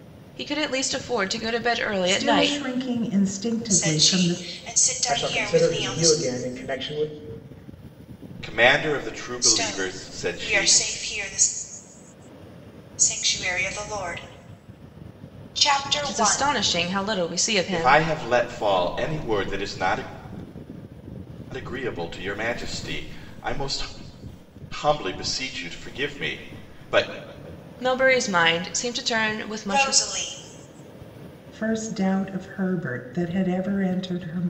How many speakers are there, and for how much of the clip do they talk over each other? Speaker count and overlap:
five, about 14%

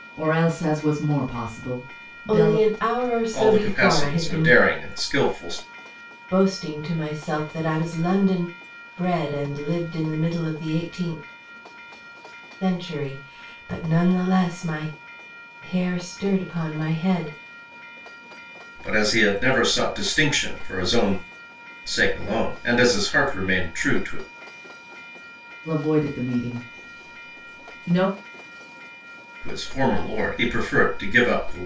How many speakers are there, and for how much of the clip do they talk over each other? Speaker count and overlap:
three, about 5%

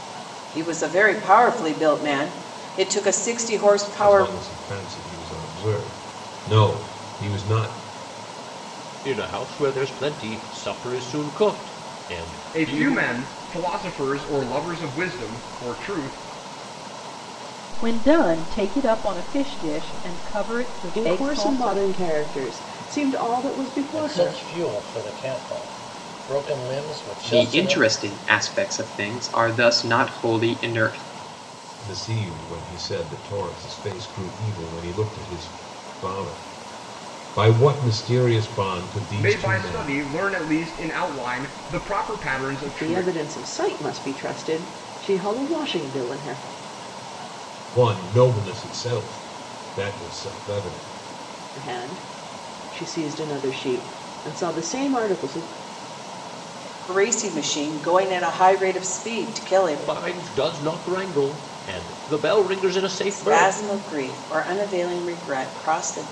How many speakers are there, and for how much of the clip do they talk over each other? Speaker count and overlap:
eight, about 9%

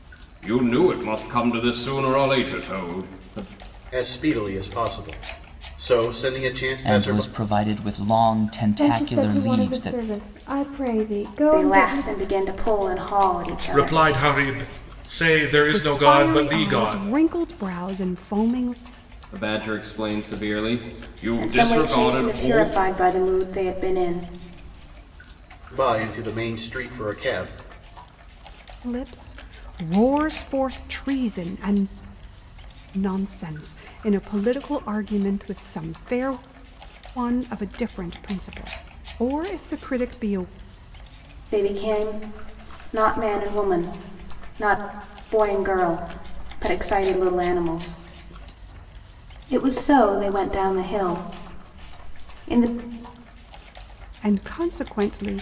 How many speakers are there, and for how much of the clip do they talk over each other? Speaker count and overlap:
seven, about 10%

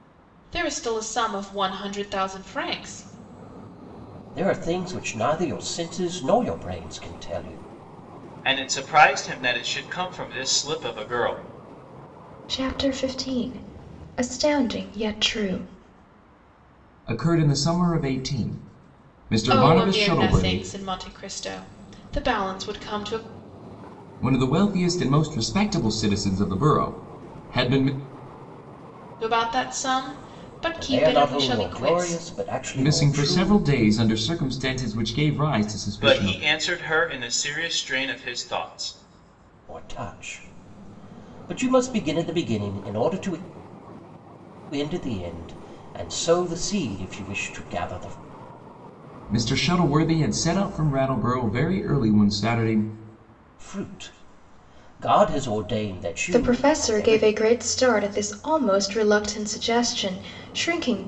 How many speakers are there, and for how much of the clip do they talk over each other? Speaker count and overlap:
five, about 8%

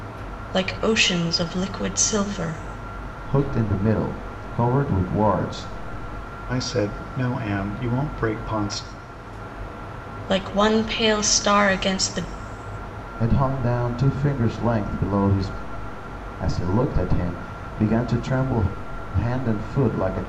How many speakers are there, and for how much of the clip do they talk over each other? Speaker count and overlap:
three, no overlap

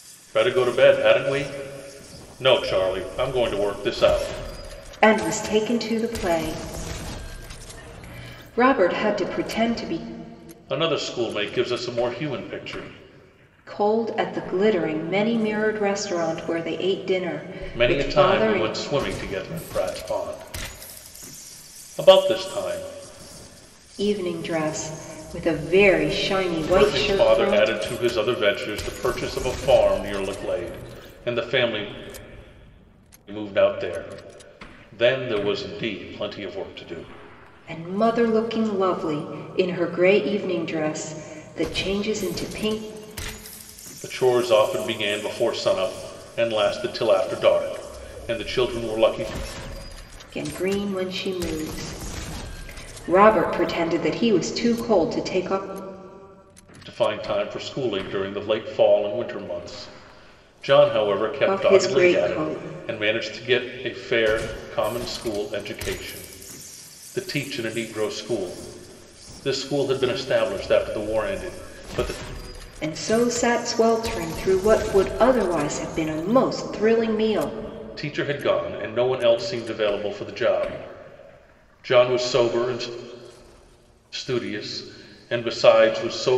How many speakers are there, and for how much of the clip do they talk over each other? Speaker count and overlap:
two, about 4%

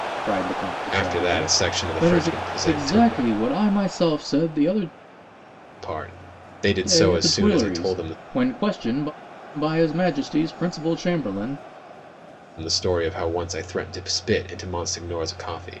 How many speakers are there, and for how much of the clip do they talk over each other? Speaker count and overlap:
two, about 22%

